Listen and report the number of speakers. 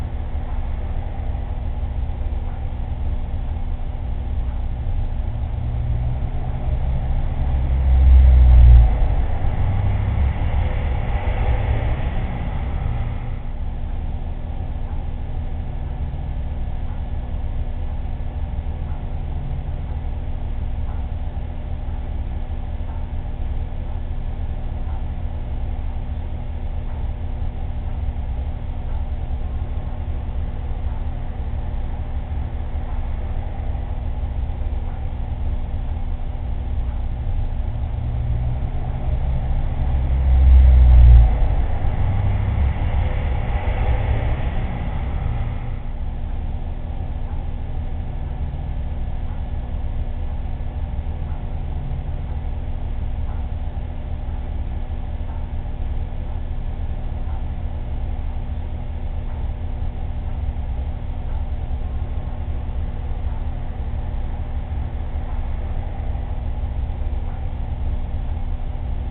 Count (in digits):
0